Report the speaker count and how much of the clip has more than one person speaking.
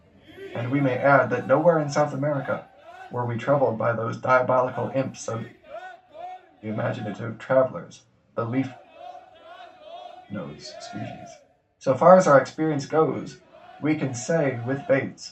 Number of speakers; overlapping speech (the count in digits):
1, no overlap